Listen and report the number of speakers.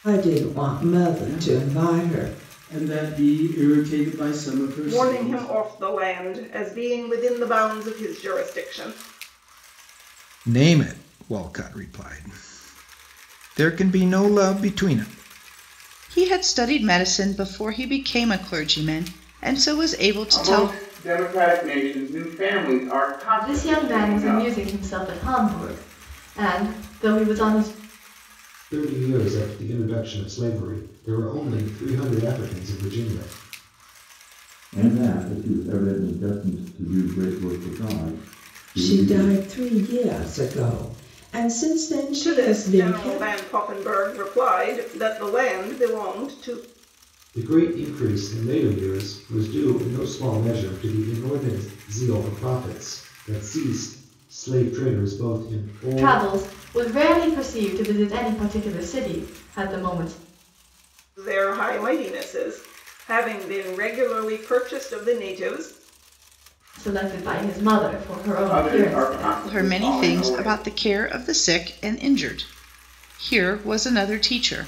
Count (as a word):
nine